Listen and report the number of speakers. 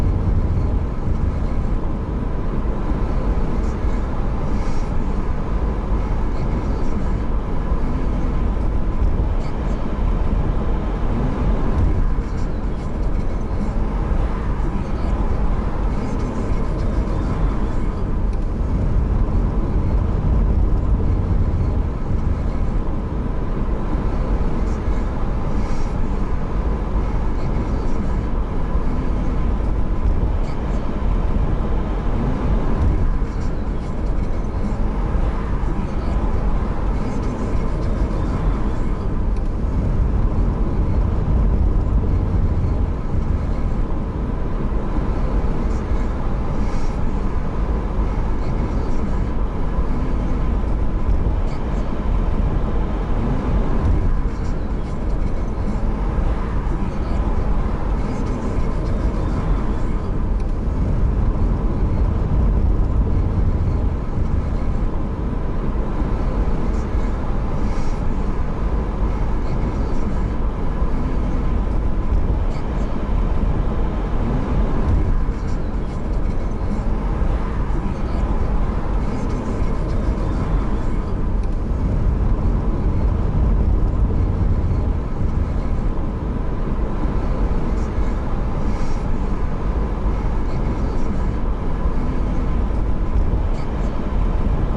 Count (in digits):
0